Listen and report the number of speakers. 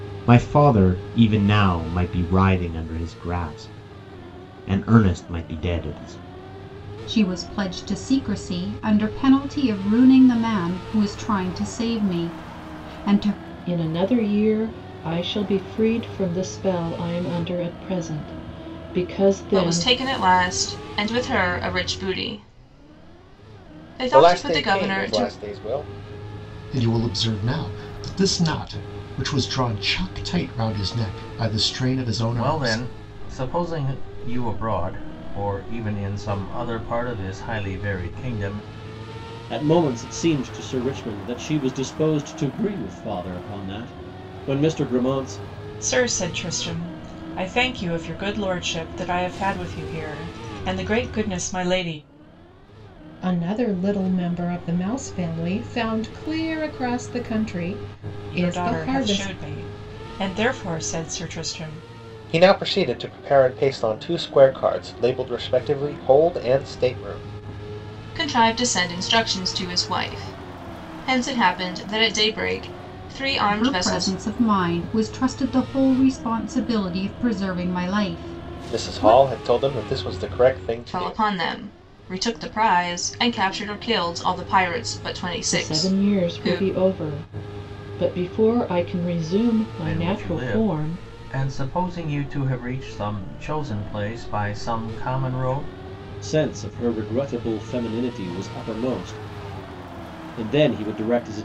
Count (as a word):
ten